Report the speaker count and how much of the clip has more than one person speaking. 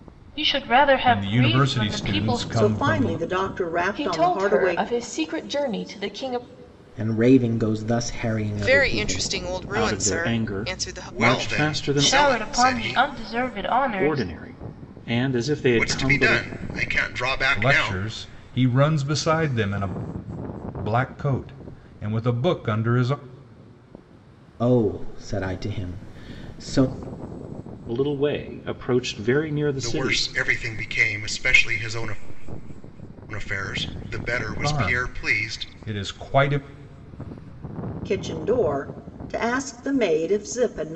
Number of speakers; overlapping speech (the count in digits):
8, about 25%